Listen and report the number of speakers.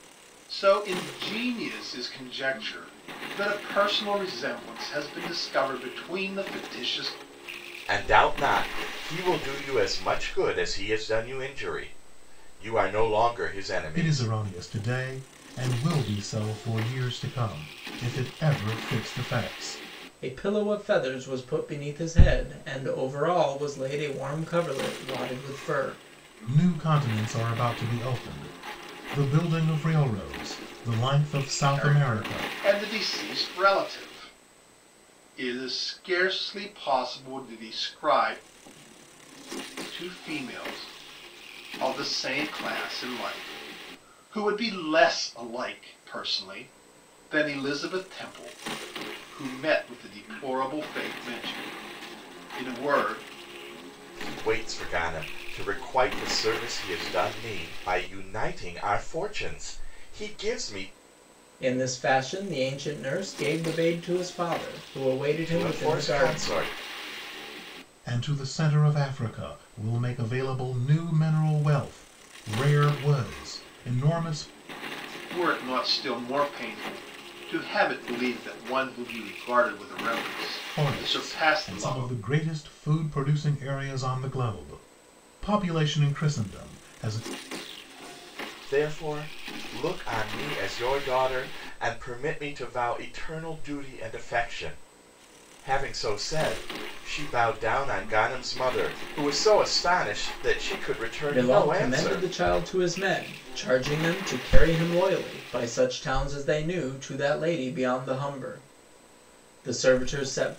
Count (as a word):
four